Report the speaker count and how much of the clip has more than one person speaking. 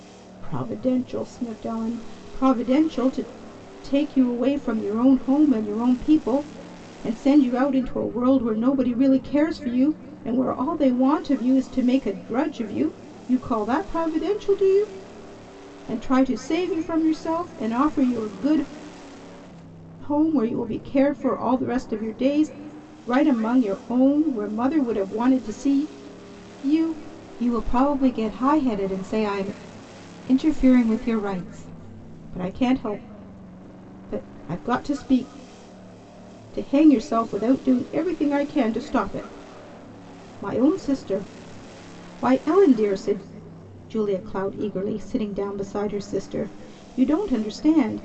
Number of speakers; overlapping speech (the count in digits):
1, no overlap